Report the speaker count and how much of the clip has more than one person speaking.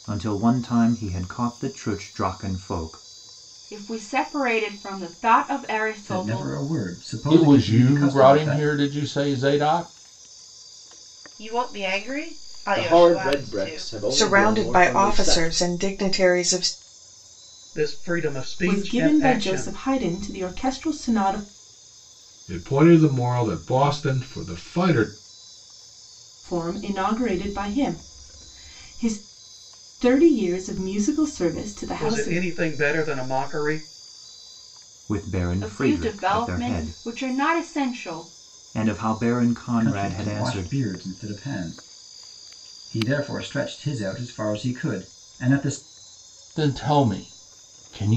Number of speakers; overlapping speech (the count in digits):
10, about 18%